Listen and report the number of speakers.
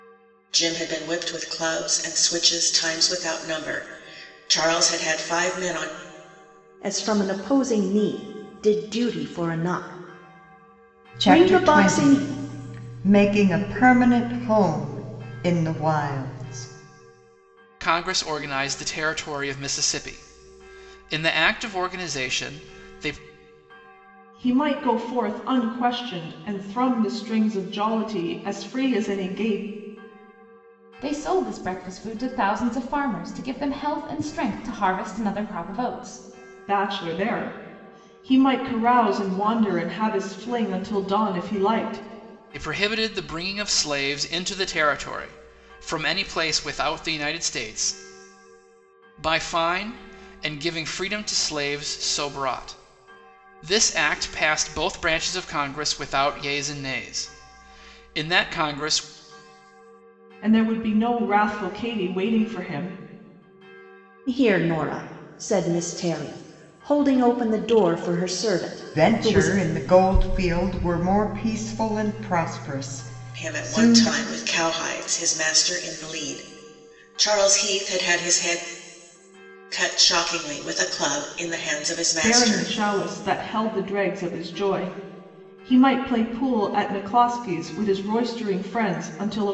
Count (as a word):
six